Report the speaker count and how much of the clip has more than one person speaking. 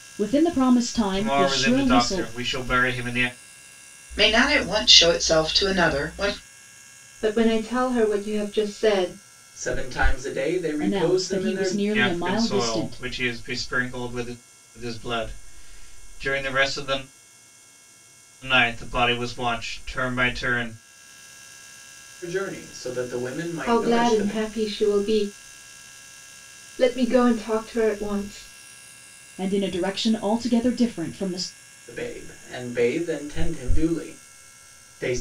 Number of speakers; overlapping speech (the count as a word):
five, about 12%